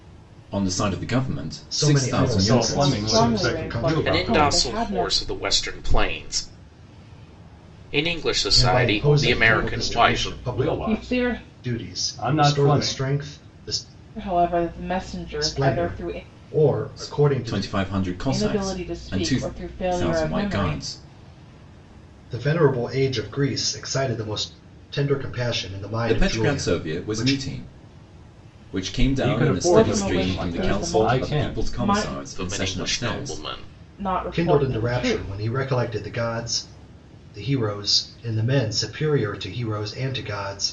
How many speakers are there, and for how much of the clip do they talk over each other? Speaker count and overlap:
5, about 44%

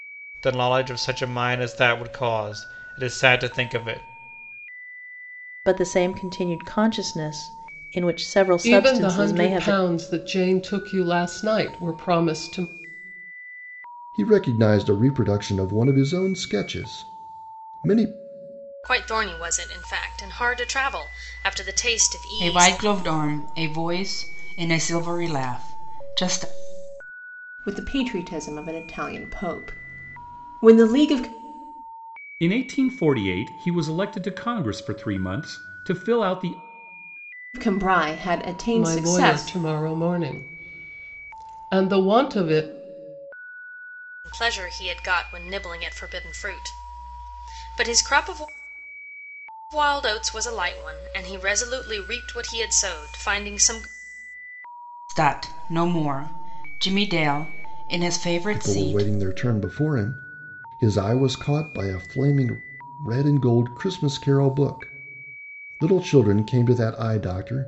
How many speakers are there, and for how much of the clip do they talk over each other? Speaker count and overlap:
8, about 5%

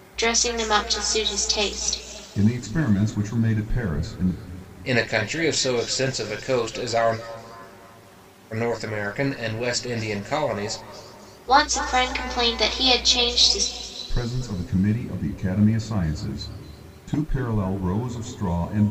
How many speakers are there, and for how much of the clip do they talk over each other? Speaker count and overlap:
3, no overlap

